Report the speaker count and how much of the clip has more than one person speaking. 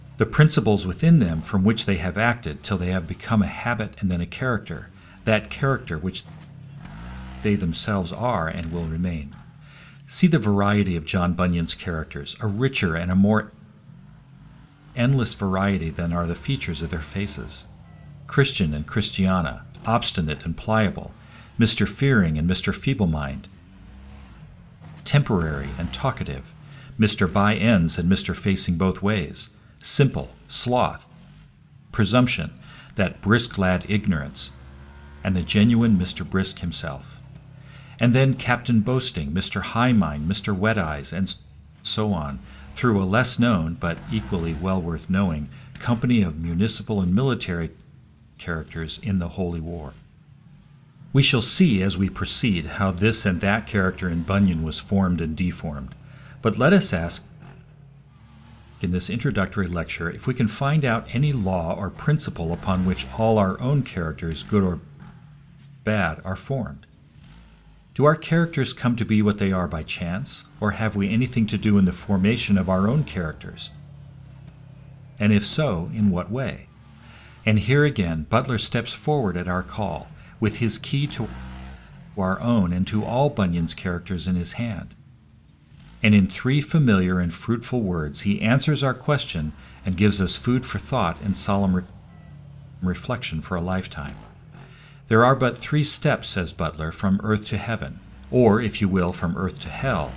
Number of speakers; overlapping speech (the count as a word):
one, no overlap